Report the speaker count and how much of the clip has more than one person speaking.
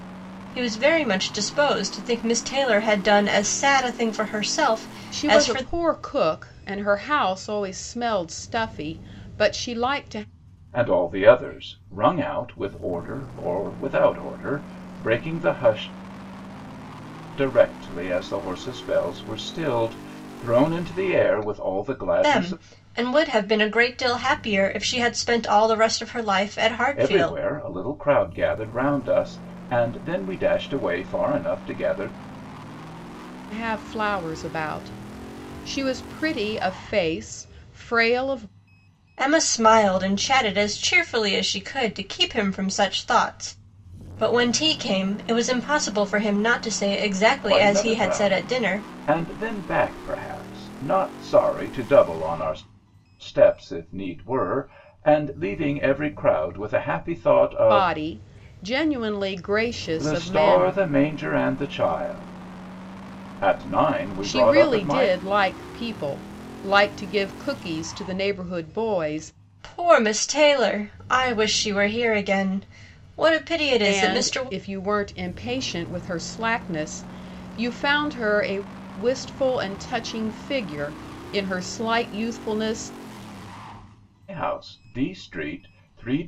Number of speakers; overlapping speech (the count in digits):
3, about 7%